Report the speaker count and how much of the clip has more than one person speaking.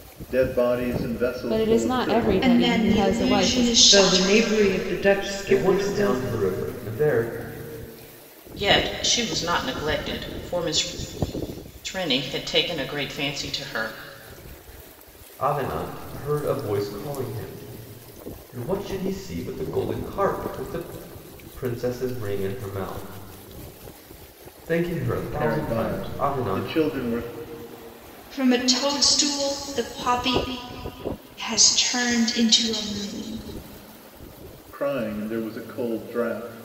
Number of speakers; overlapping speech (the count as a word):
six, about 14%